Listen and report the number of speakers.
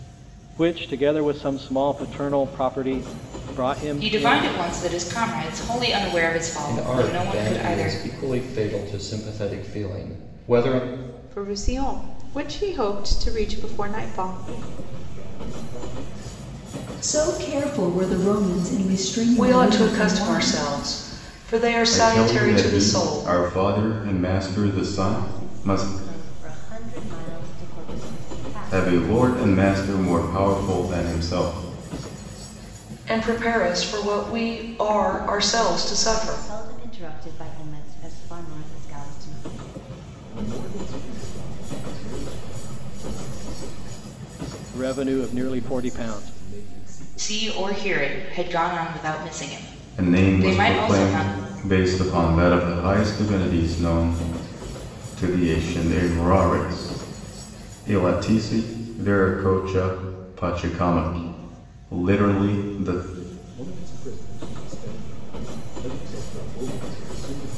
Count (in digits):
9